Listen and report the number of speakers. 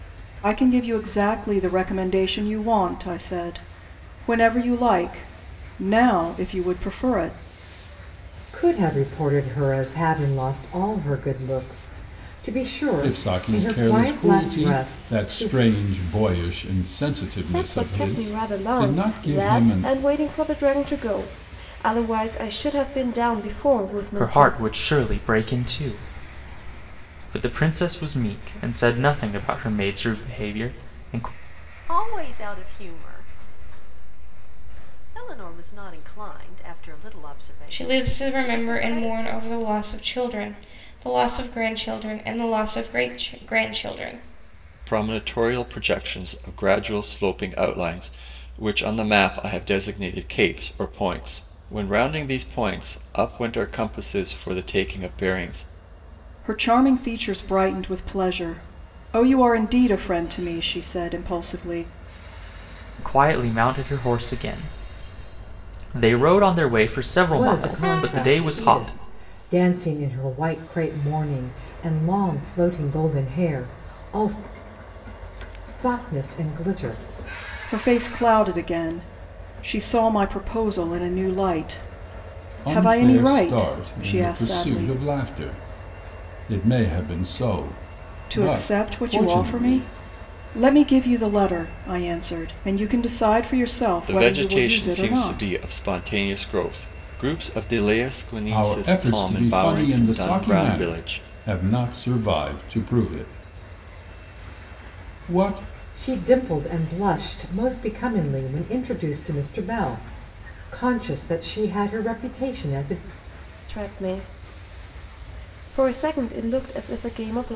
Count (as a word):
eight